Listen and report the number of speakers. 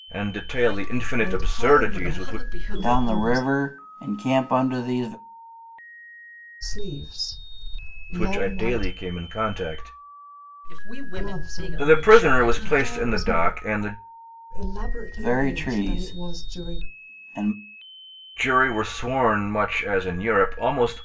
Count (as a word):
four